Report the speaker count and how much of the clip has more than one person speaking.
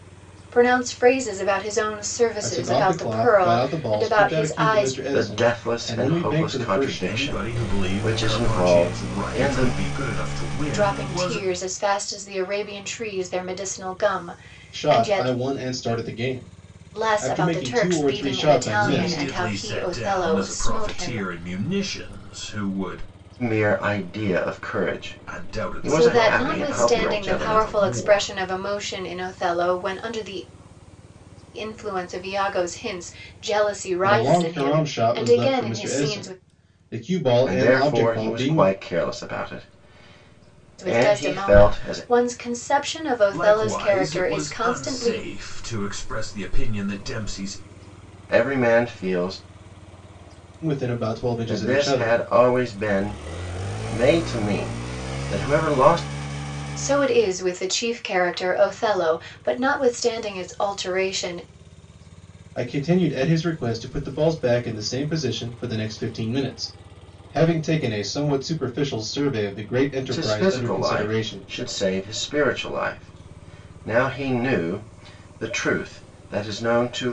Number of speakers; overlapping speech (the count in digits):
4, about 32%